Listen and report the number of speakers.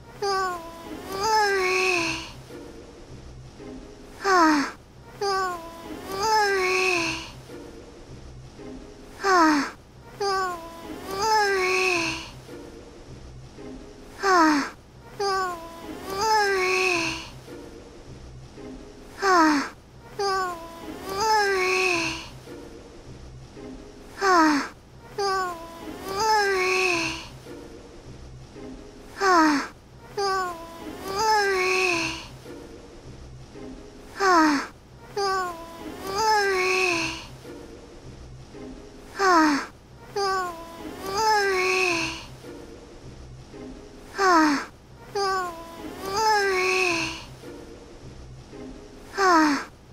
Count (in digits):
0